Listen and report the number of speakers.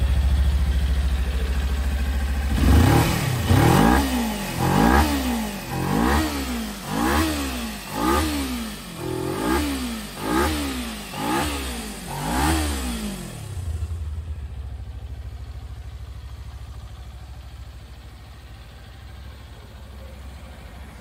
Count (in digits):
0